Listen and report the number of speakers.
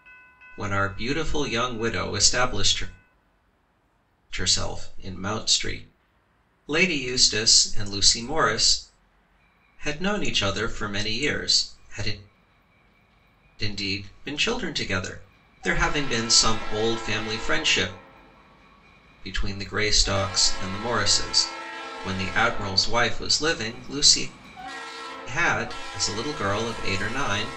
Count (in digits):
1